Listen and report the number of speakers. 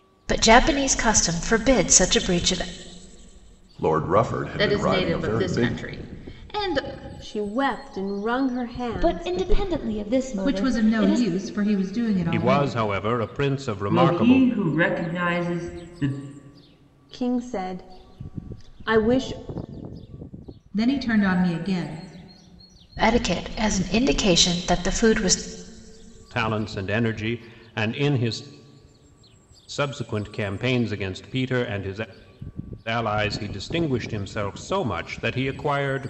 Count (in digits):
8